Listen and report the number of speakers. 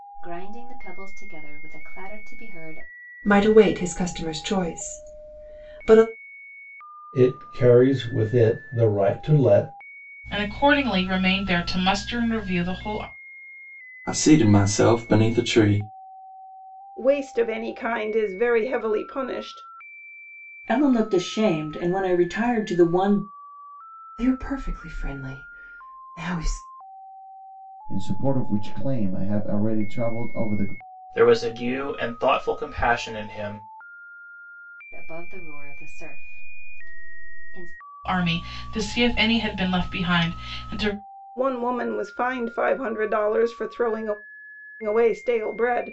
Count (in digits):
10